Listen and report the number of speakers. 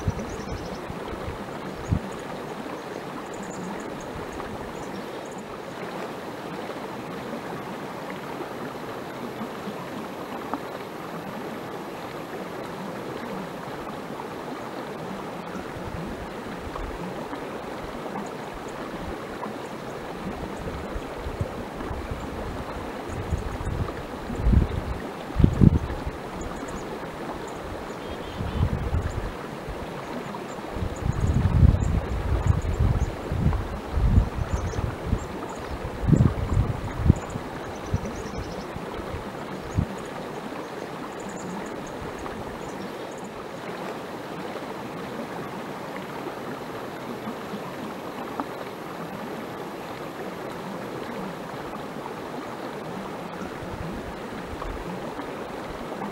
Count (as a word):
zero